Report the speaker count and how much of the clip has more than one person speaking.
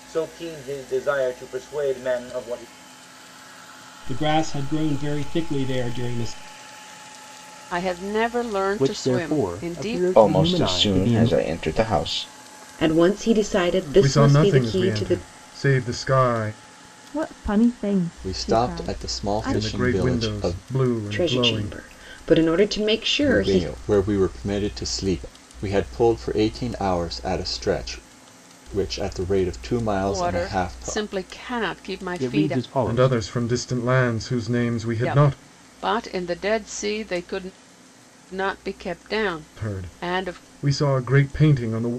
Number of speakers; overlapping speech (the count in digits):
9, about 25%